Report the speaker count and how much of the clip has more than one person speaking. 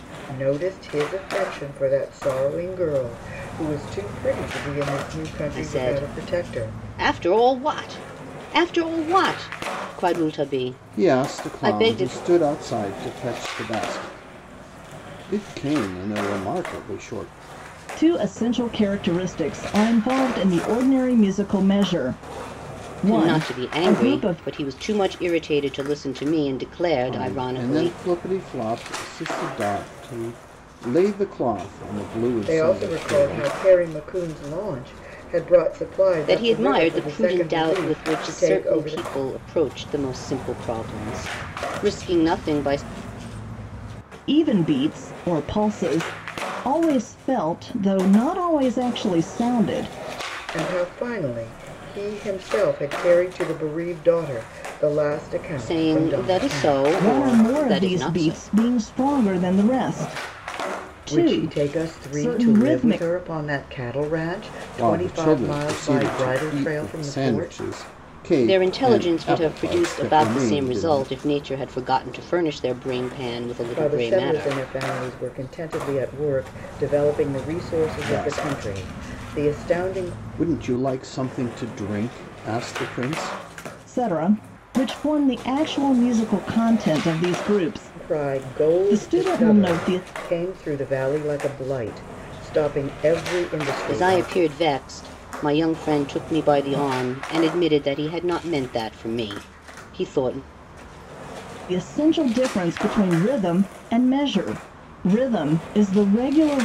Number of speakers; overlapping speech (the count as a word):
four, about 23%